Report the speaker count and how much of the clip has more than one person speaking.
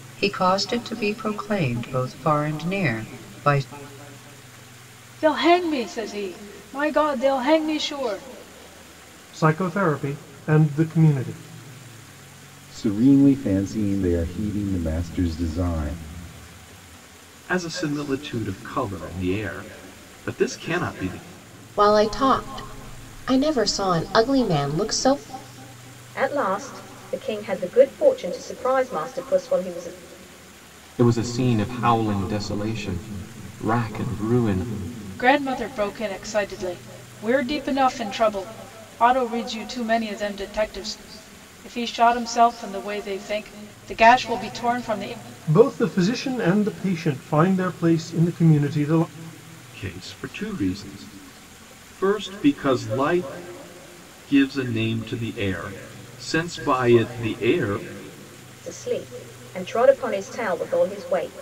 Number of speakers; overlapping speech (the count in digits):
8, no overlap